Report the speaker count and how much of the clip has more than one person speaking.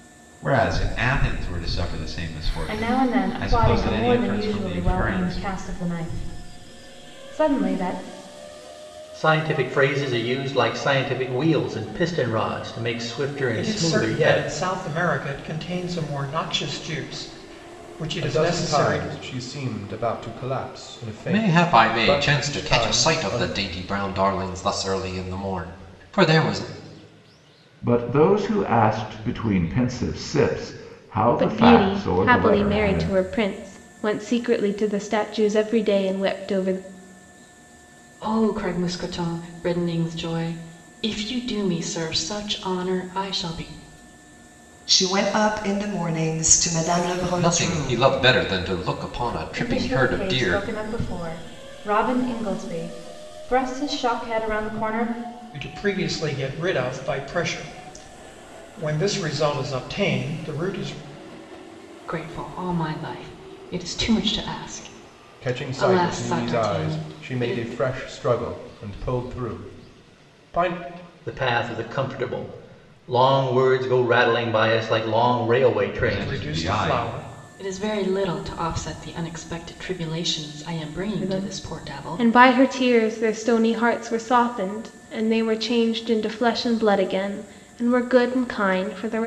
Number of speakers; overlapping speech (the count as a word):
ten, about 17%